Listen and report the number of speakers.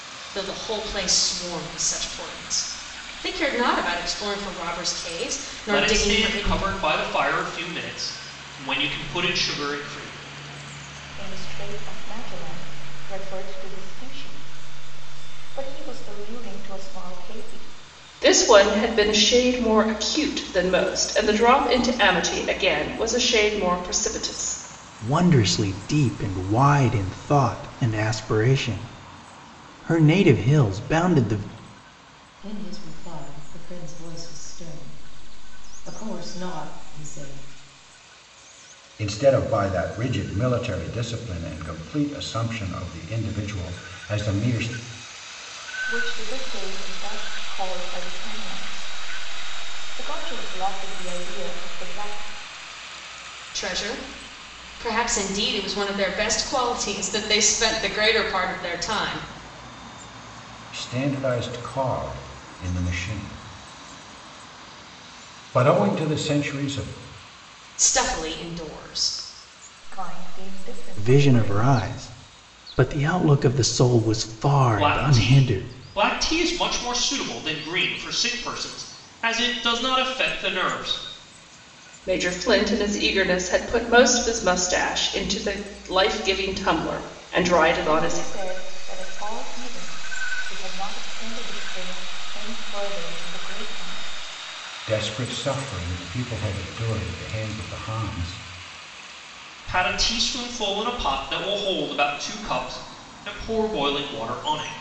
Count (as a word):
seven